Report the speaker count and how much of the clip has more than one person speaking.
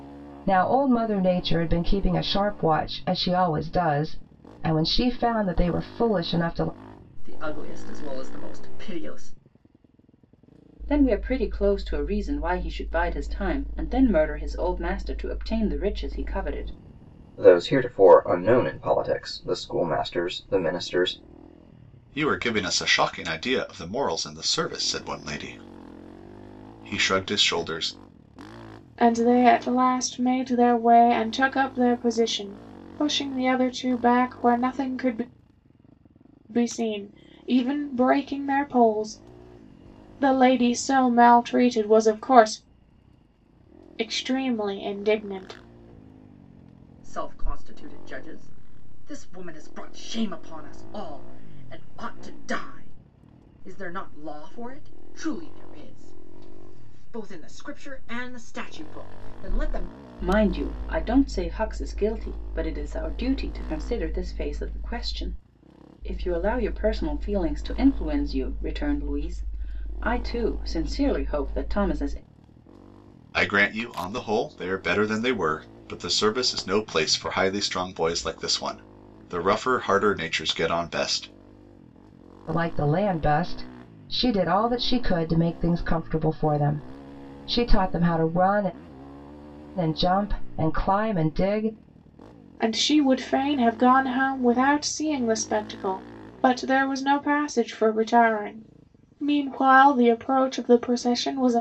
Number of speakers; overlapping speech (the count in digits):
6, no overlap